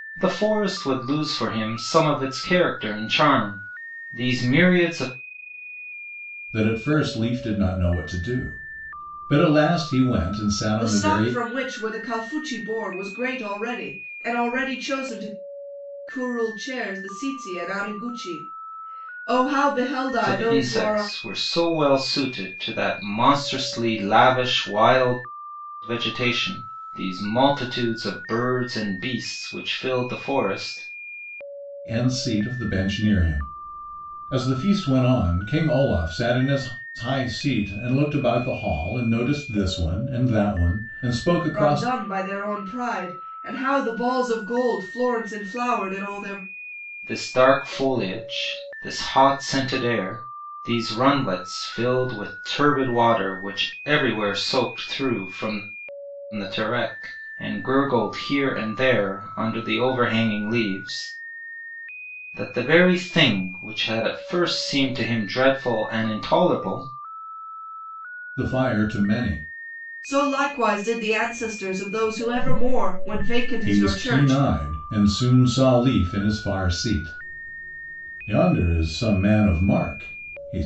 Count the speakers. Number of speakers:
3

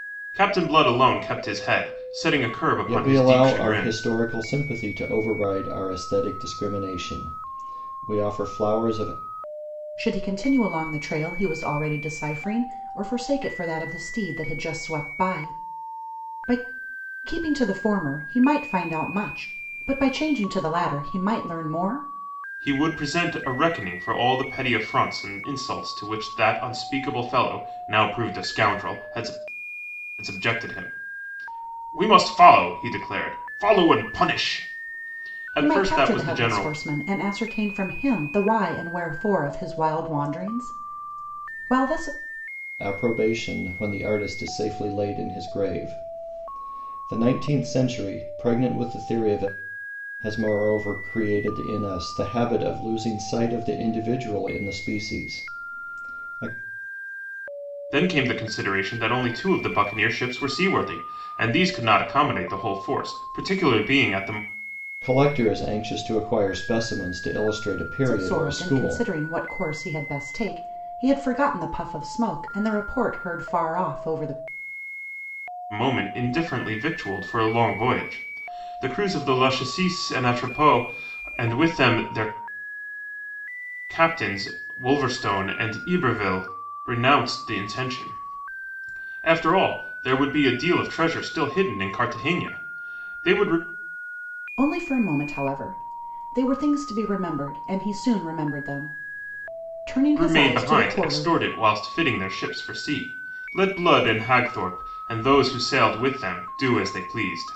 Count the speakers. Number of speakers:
3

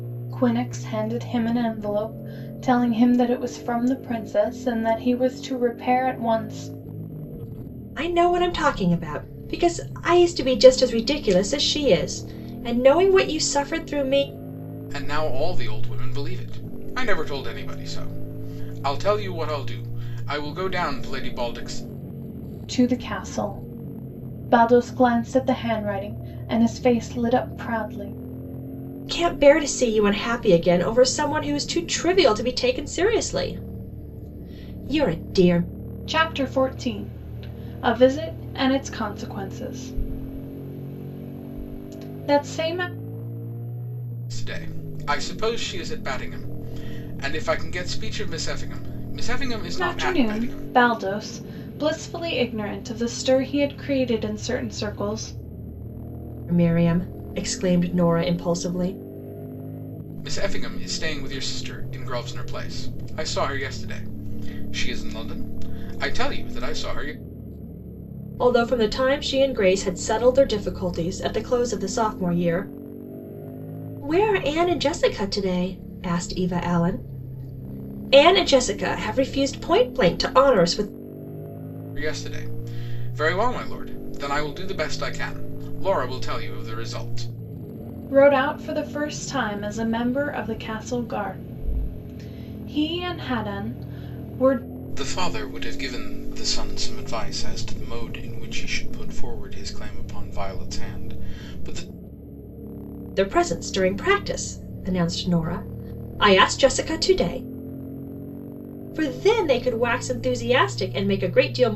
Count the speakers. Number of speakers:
3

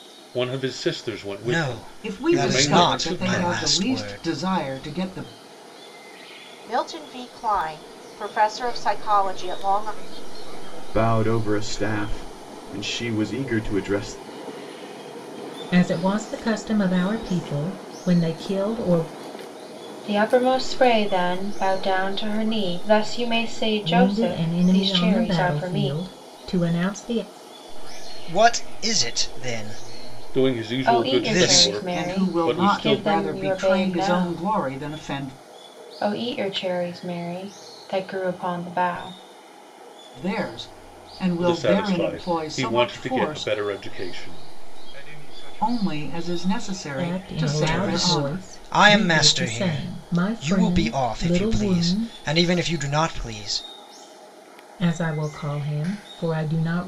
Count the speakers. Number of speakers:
8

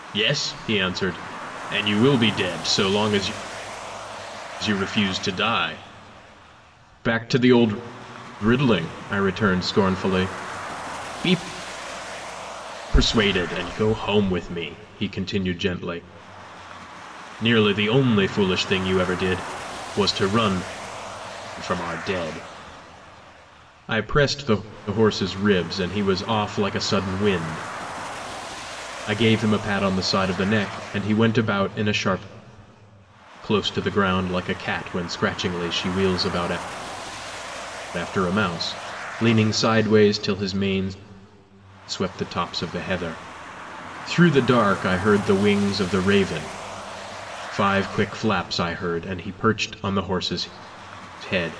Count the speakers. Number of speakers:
1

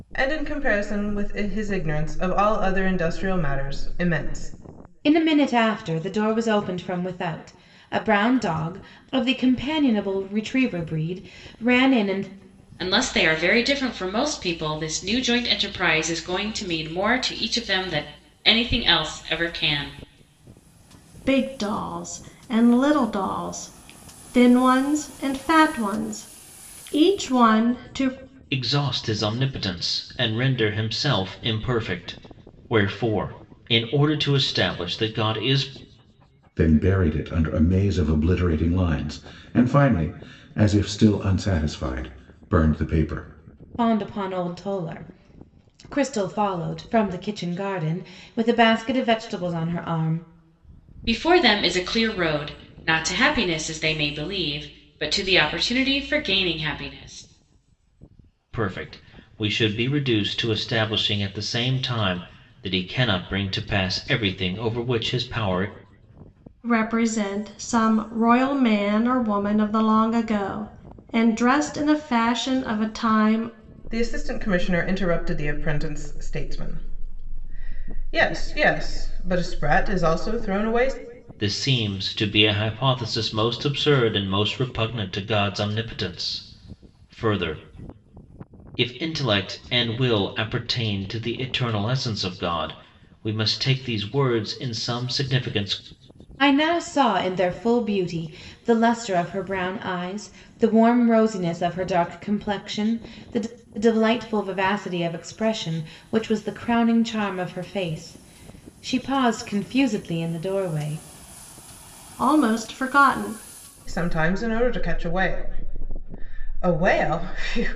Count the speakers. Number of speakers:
6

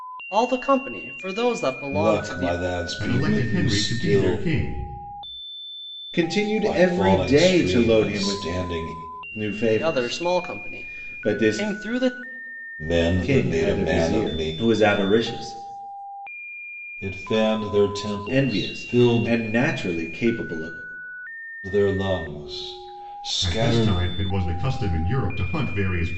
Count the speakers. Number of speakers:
4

